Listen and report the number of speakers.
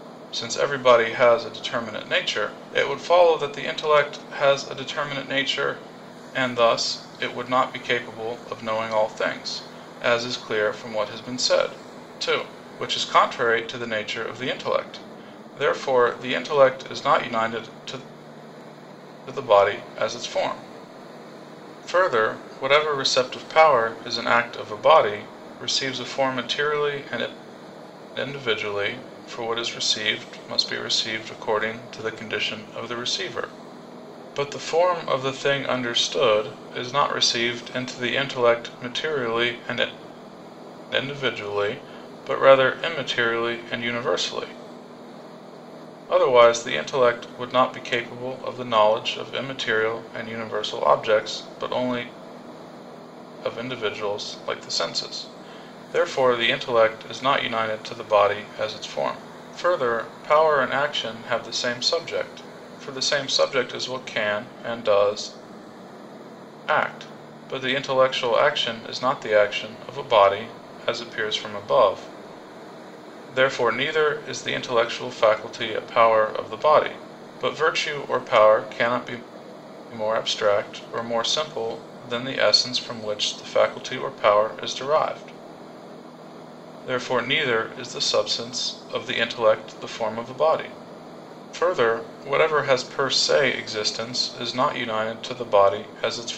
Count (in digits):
1